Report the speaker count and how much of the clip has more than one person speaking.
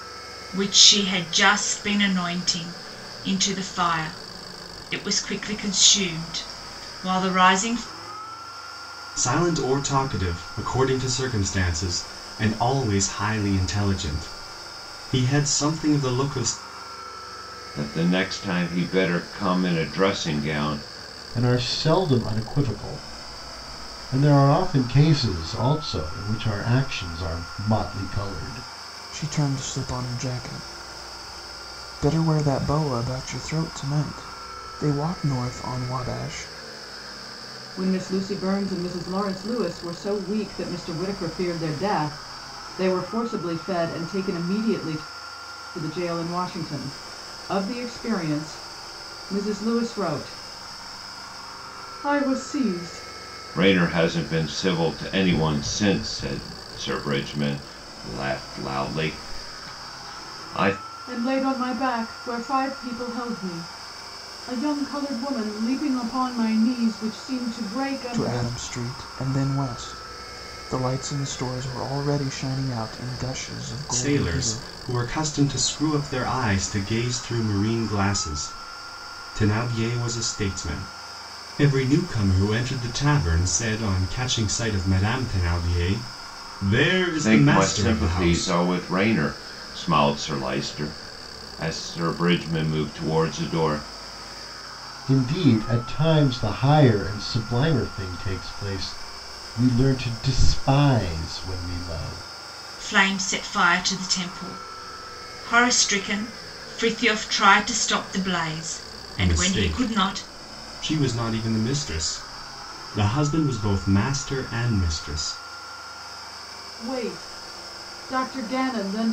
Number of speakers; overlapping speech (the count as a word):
six, about 3%